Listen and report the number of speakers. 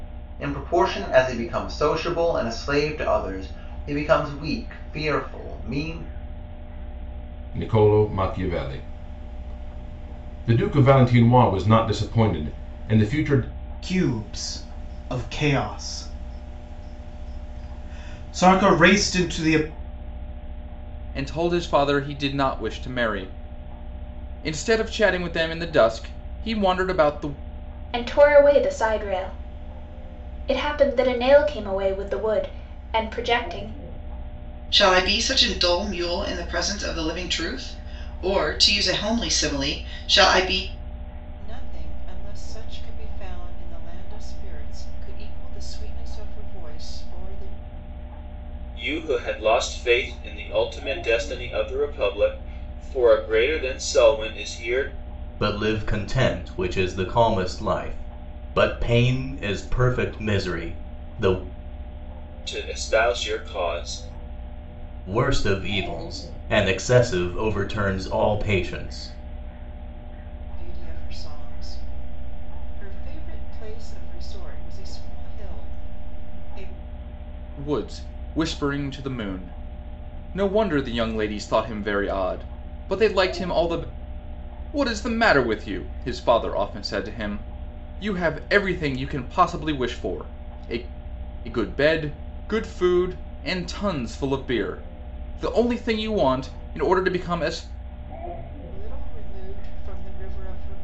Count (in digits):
9